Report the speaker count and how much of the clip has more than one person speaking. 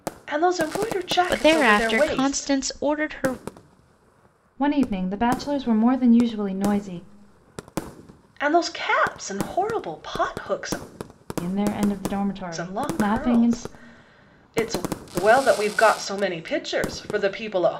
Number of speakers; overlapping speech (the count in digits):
3, about 14%